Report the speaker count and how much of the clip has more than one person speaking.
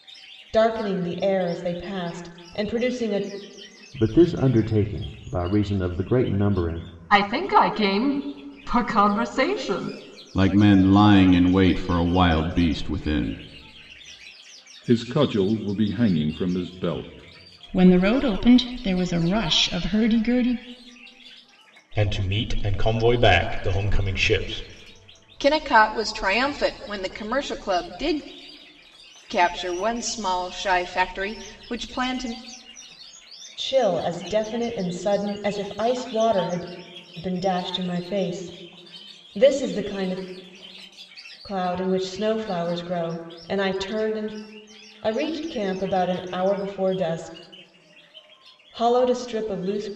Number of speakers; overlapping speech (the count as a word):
eight, no overlap